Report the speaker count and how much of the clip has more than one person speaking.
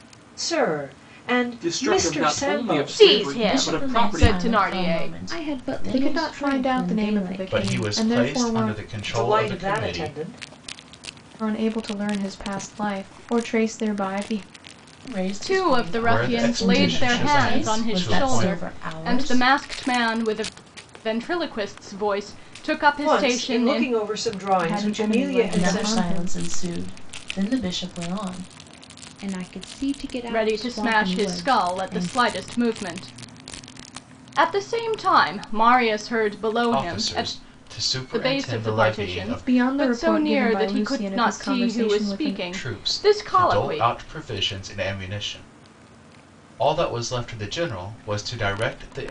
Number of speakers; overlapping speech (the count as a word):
seven, about 47%